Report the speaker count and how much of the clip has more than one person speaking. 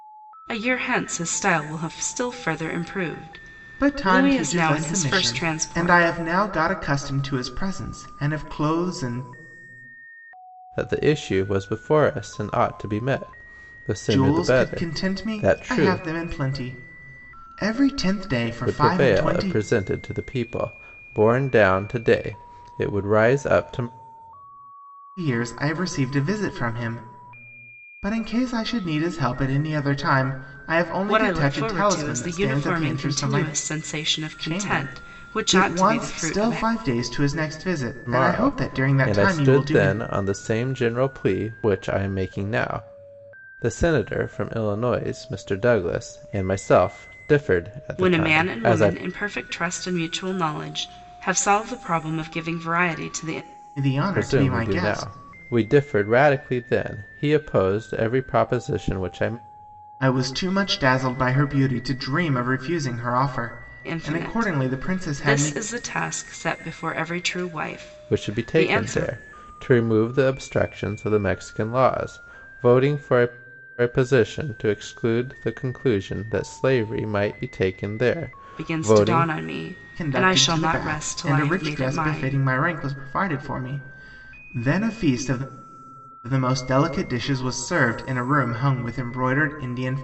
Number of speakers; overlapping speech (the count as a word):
three, about 23%